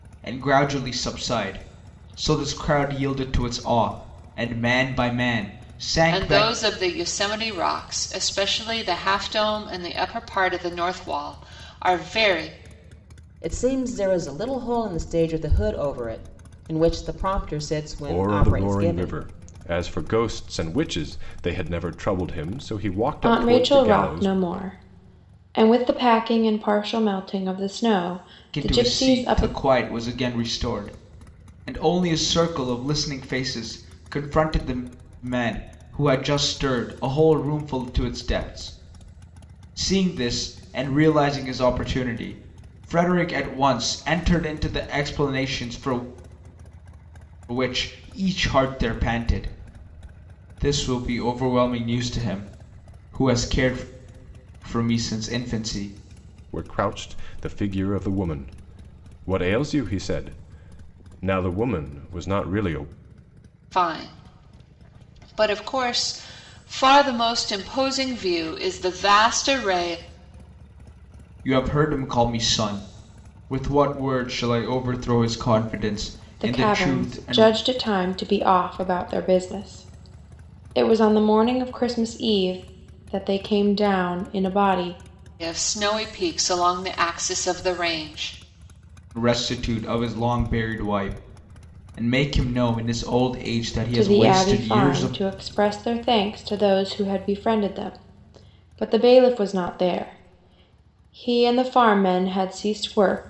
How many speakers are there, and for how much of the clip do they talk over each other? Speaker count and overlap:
five, about 6%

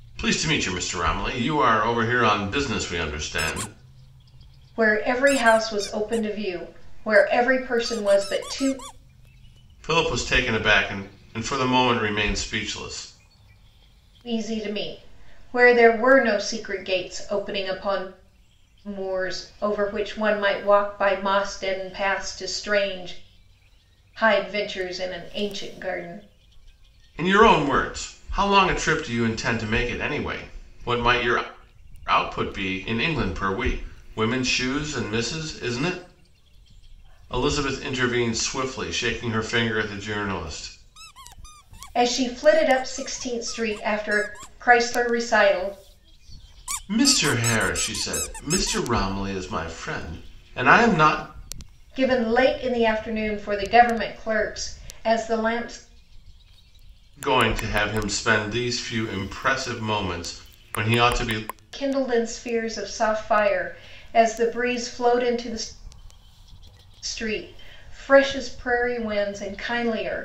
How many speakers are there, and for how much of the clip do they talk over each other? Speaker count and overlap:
two, no overlap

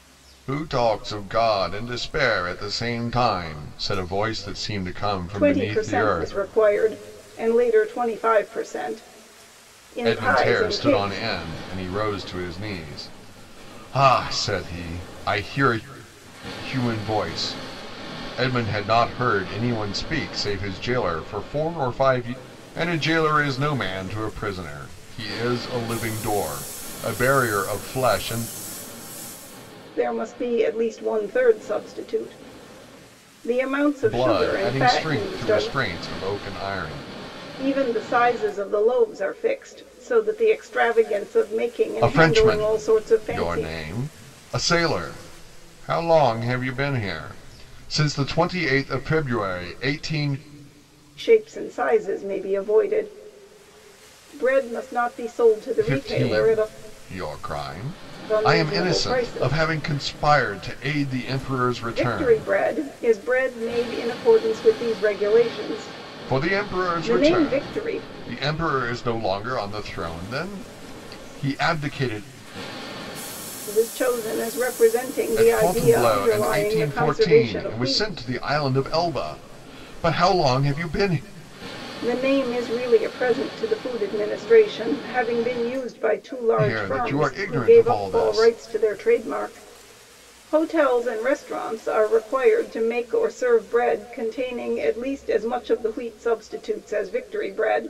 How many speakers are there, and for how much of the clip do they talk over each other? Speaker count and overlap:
two, about 16%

